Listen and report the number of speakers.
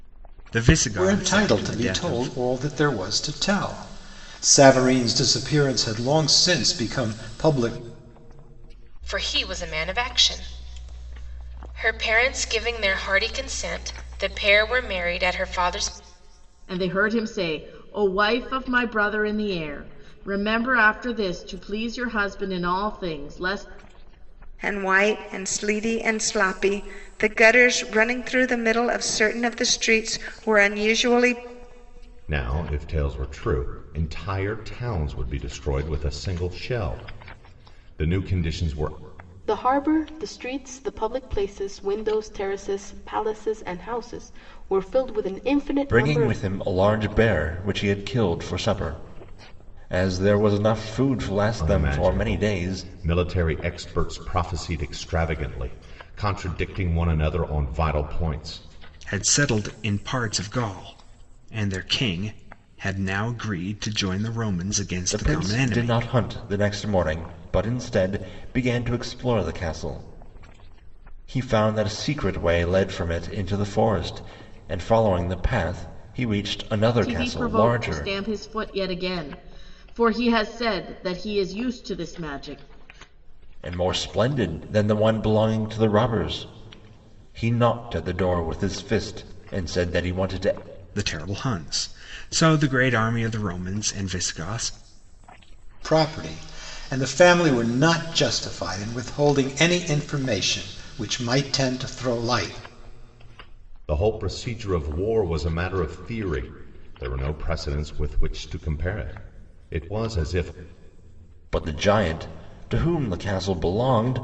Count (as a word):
eight